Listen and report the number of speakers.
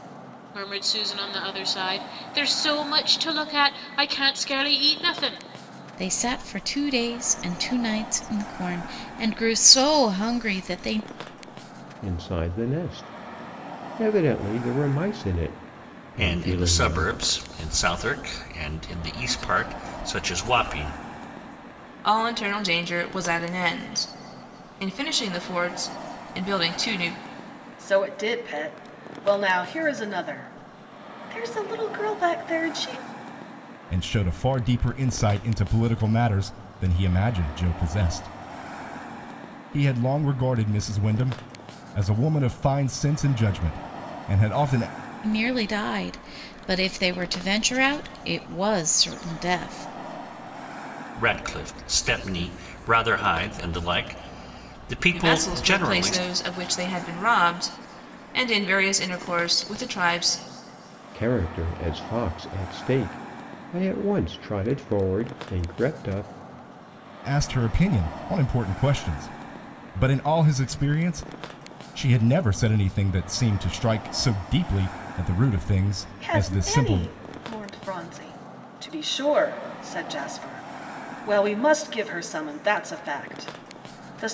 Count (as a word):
seven